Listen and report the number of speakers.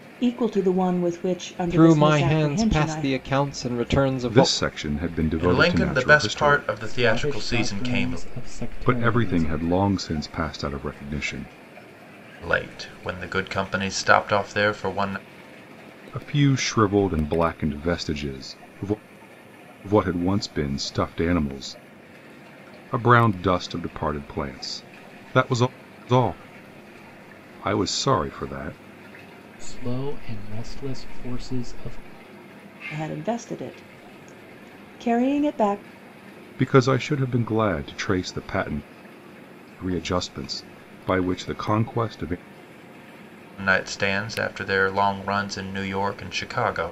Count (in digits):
5